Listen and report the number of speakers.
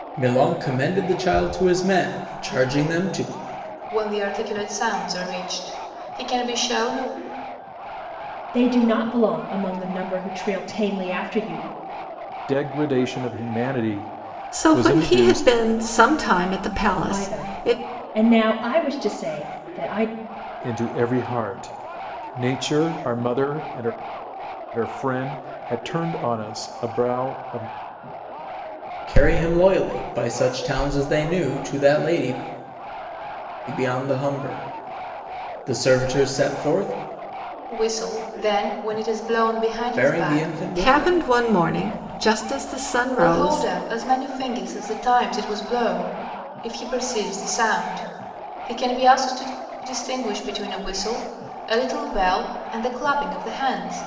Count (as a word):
five